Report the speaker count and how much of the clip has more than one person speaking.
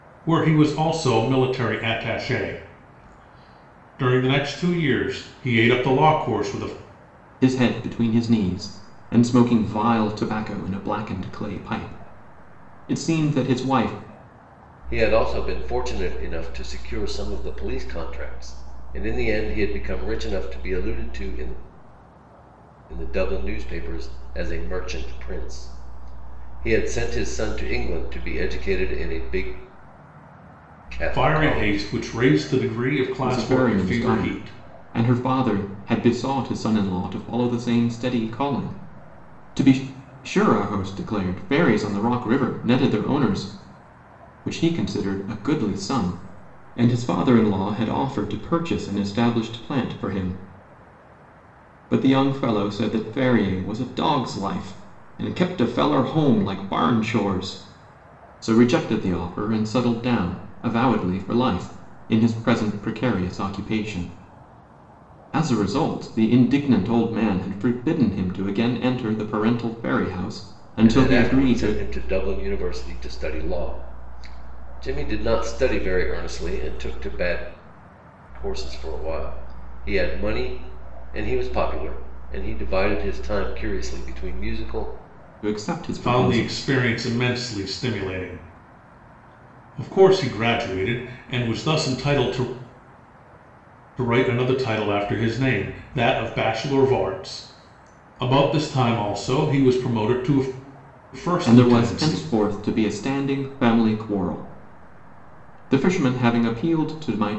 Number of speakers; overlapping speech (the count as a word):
three, about 4%